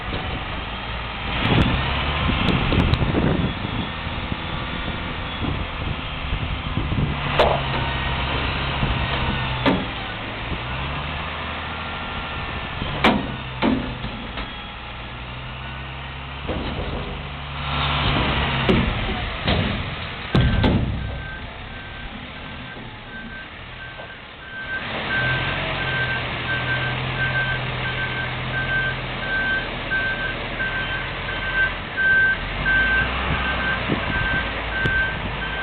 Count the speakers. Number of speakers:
0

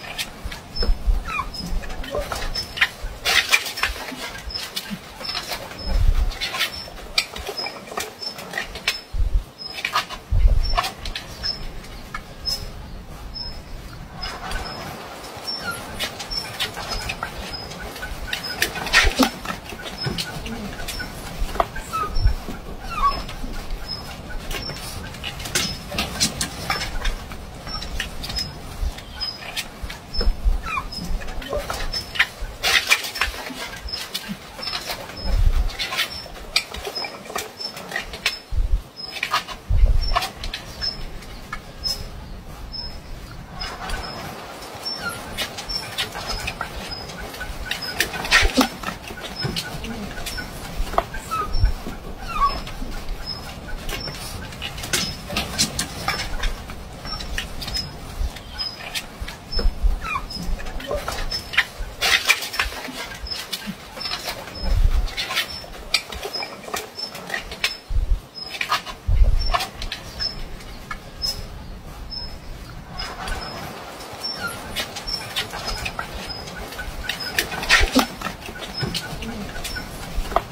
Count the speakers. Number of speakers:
0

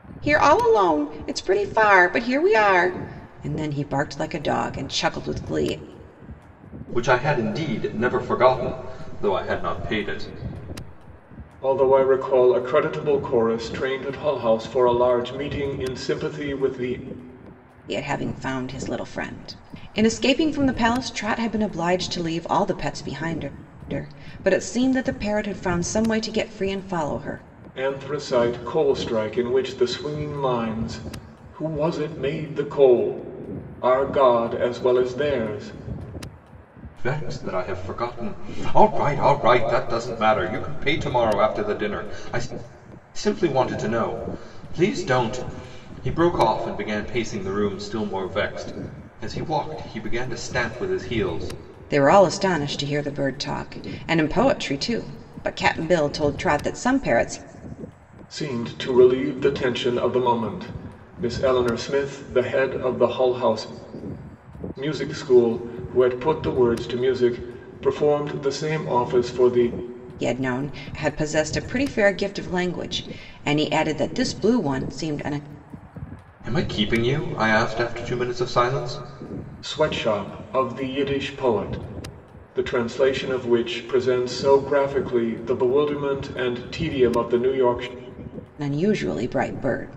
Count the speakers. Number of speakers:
3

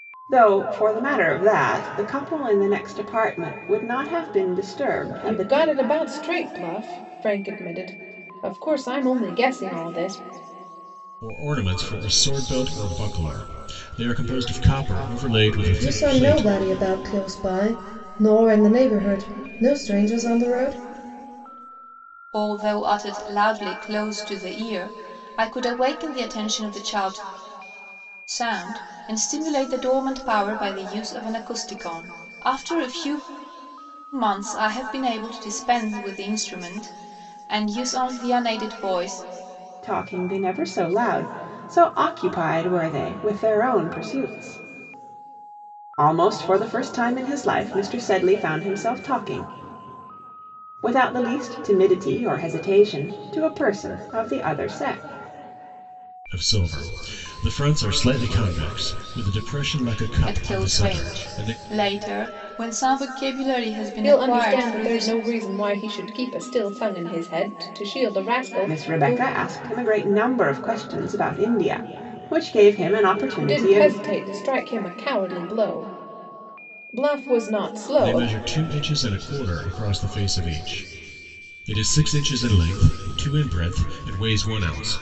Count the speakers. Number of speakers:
5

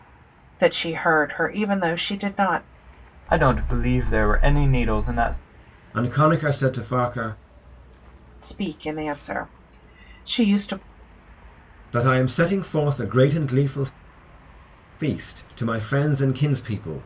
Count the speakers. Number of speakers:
3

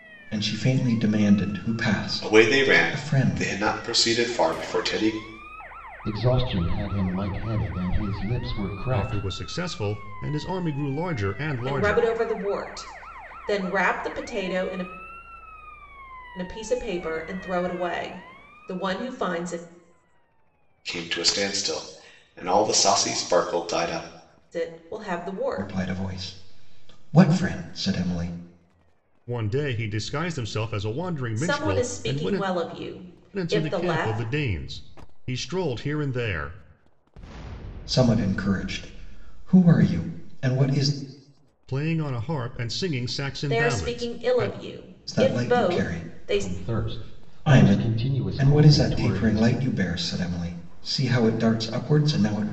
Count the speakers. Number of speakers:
5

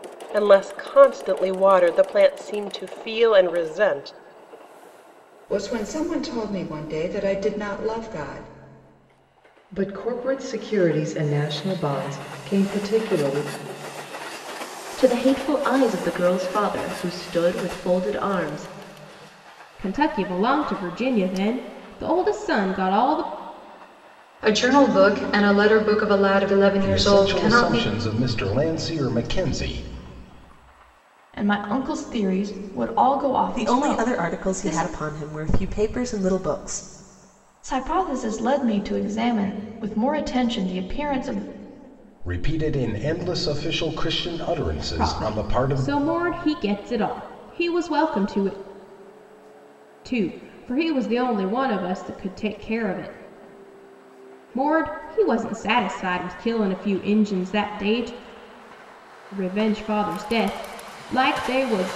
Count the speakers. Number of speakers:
9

